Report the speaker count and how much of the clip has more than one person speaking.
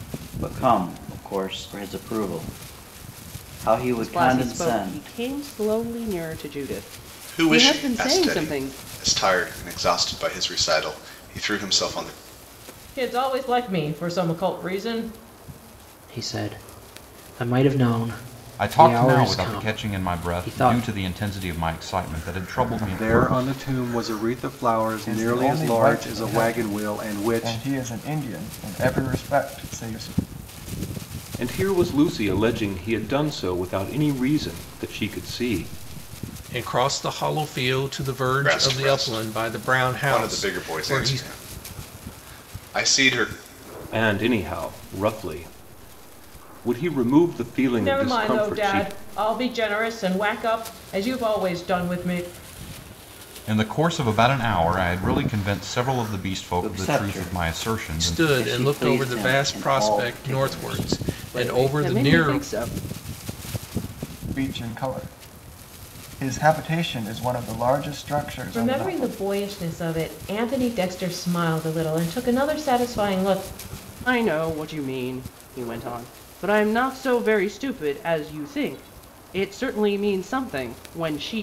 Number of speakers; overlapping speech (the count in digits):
10, about 23%